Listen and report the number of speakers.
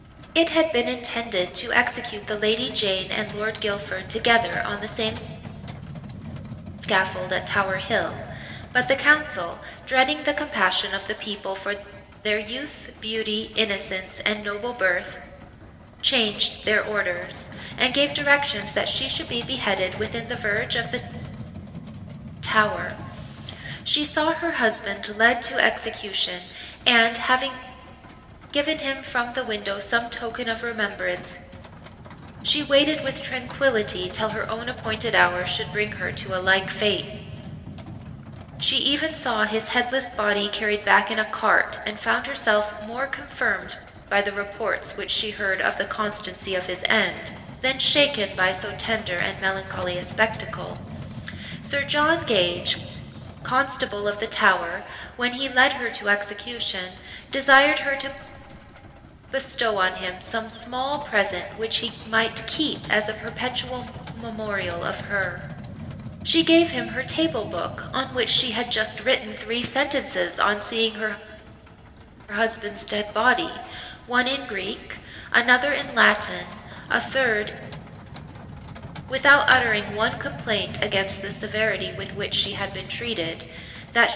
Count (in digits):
1